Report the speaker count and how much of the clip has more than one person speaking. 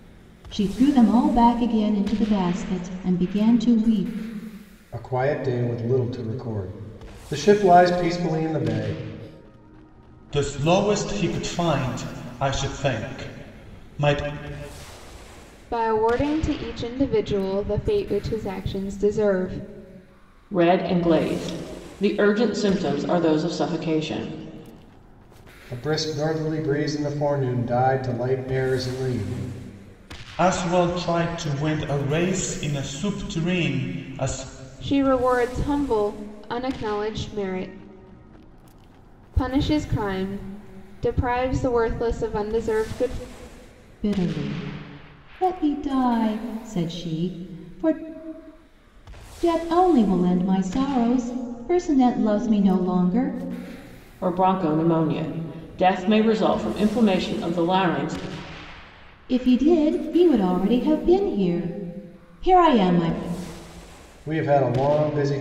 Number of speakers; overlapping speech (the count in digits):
5, no overlap